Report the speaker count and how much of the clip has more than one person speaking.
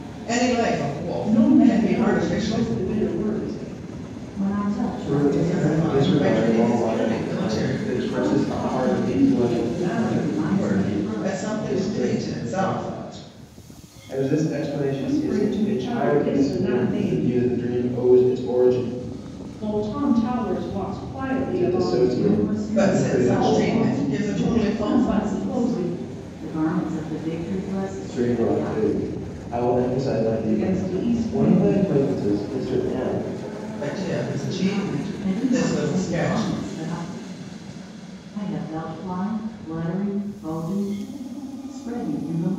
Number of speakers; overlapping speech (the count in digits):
4, about 47%